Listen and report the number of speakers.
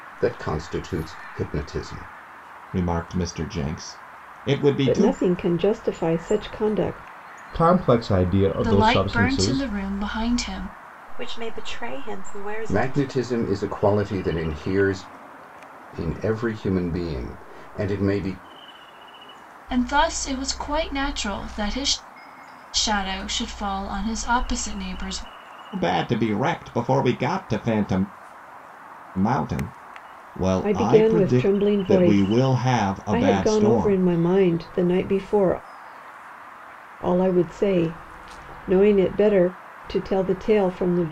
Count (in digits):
6